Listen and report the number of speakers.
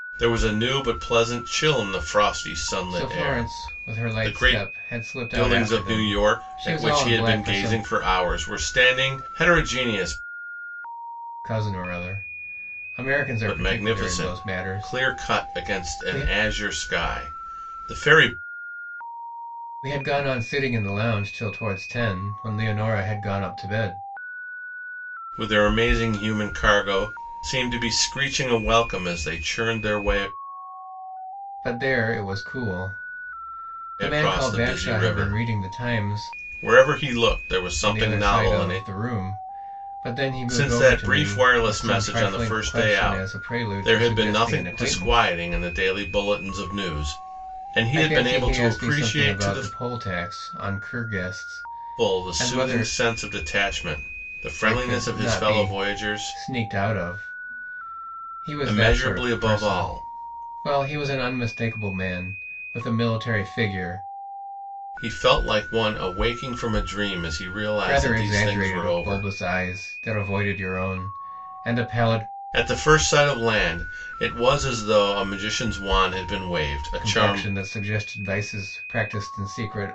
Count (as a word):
two